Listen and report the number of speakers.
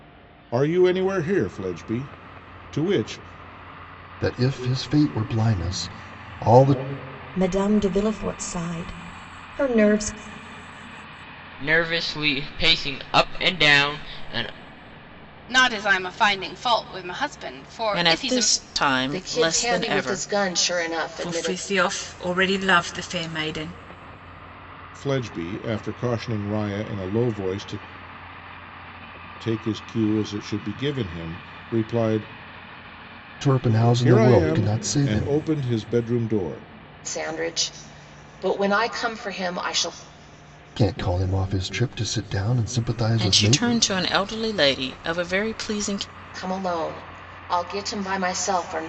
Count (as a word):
eight